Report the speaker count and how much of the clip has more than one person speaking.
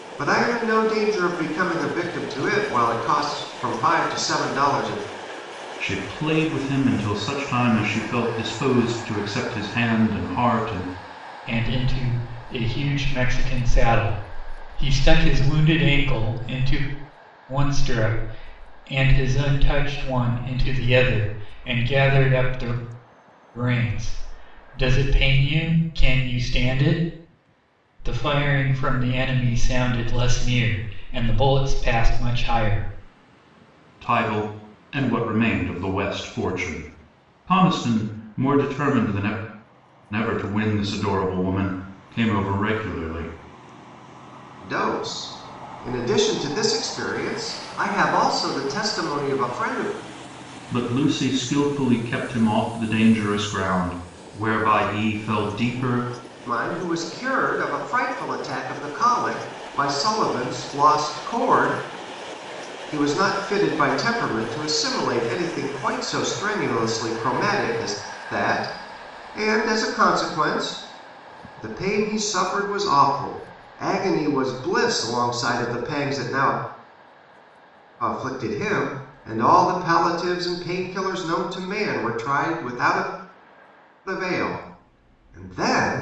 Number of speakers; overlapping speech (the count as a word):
three, no overlap